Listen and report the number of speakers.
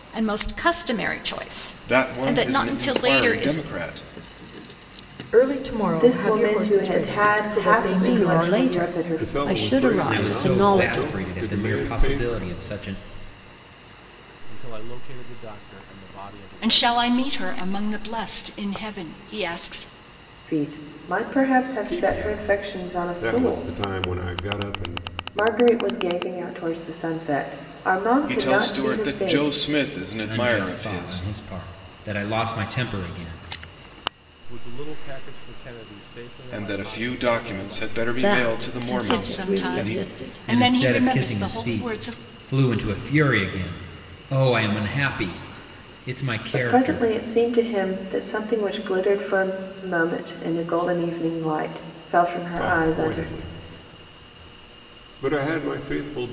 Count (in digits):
9